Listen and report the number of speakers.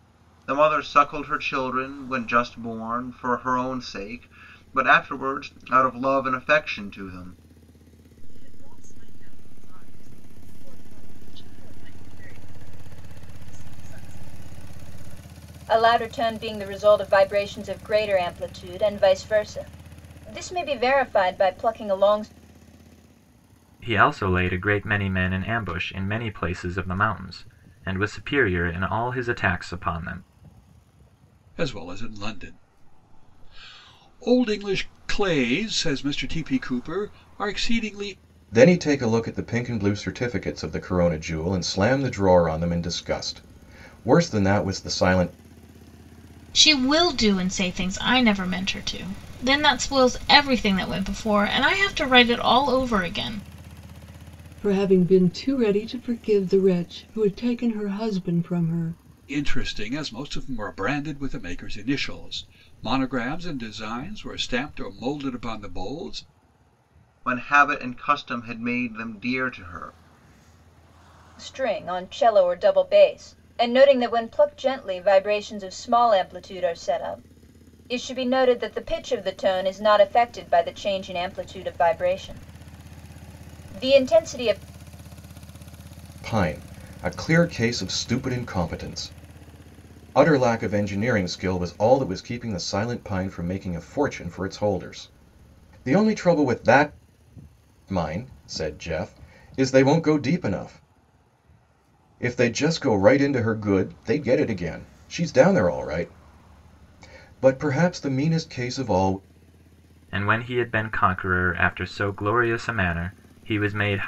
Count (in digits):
8